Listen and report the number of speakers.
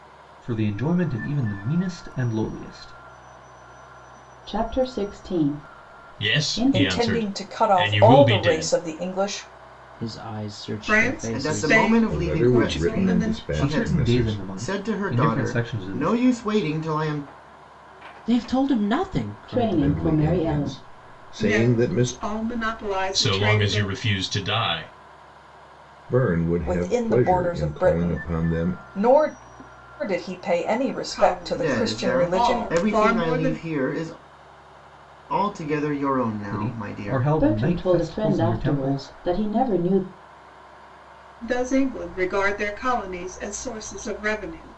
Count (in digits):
8